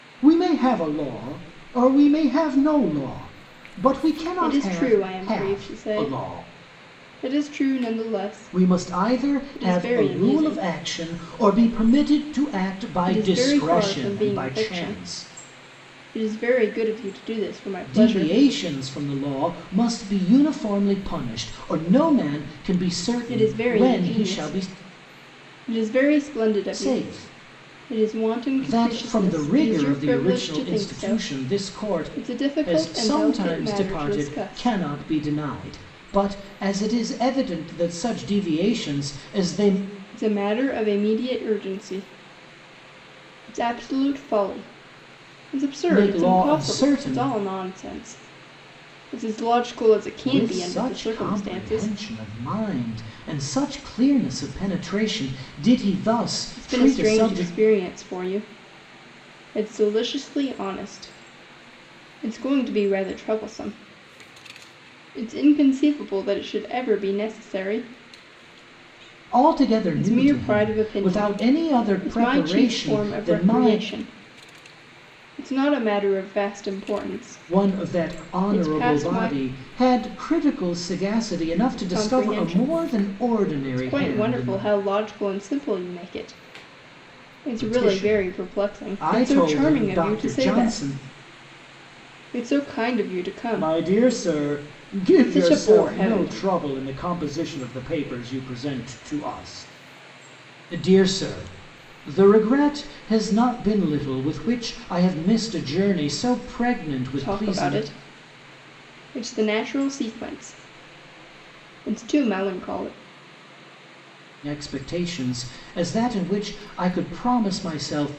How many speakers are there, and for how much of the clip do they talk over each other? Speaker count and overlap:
two, about 30%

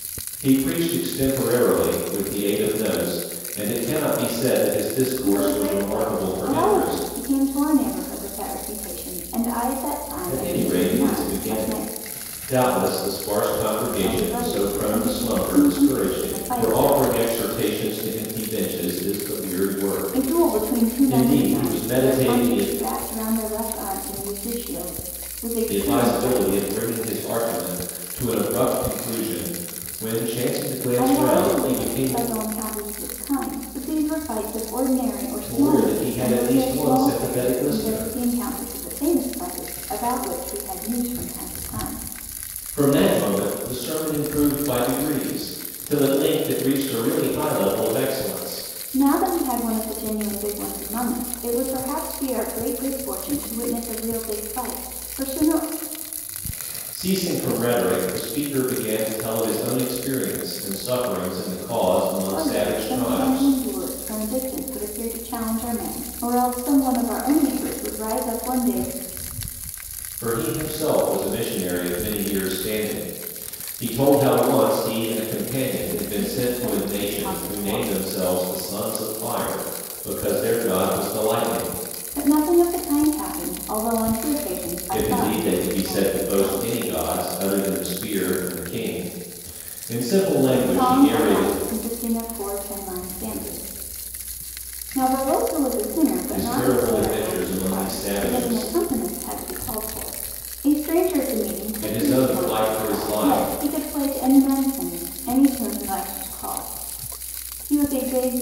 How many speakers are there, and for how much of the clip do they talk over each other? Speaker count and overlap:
two, about 23%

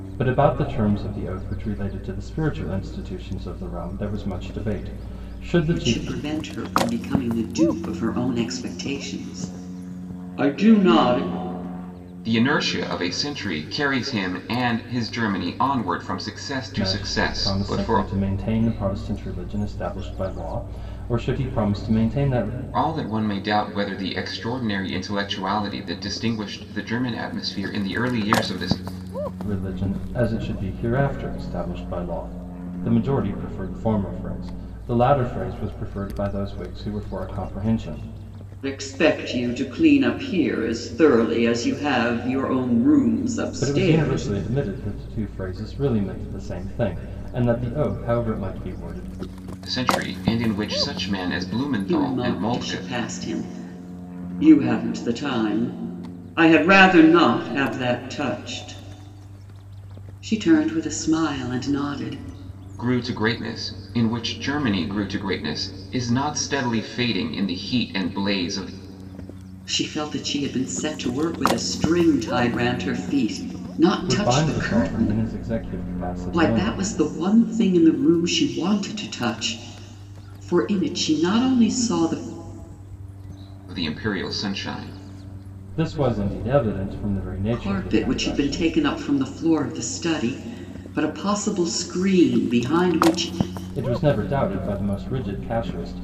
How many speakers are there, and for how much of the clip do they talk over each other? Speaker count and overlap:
three, about 7%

